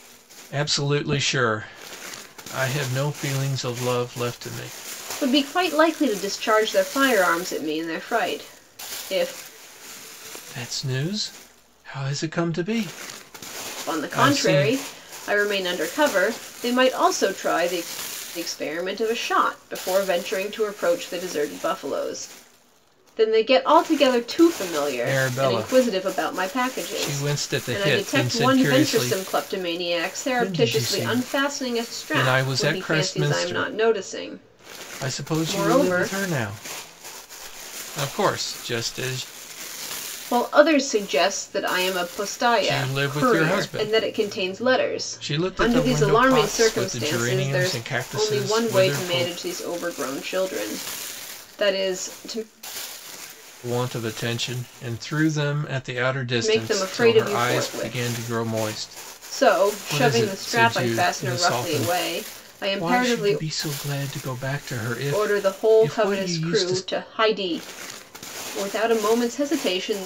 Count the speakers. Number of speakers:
two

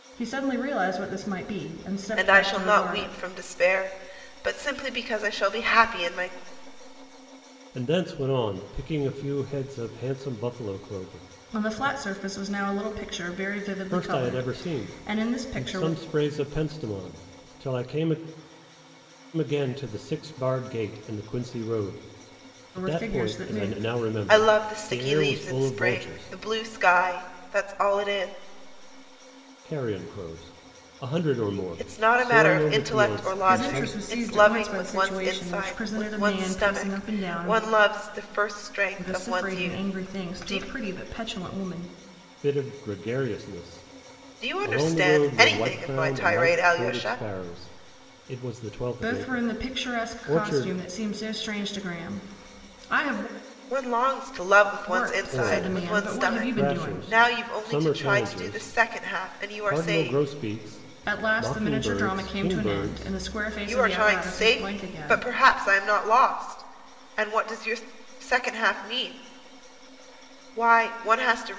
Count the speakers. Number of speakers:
three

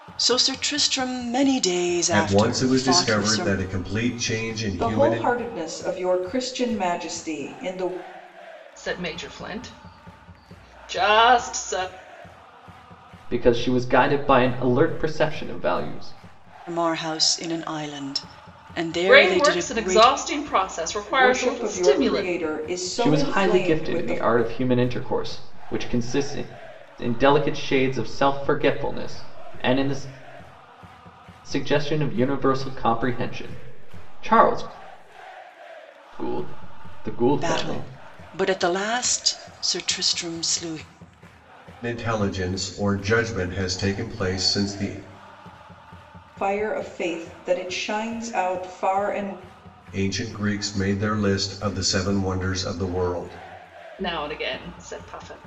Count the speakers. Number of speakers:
five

